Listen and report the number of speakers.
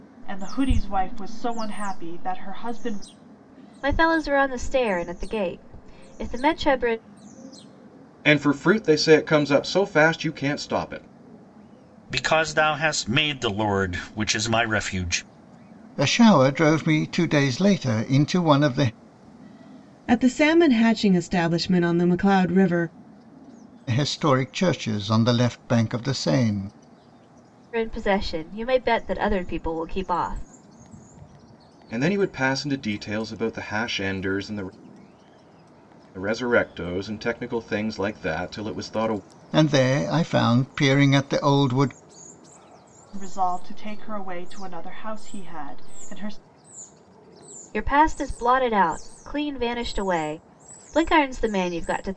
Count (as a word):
six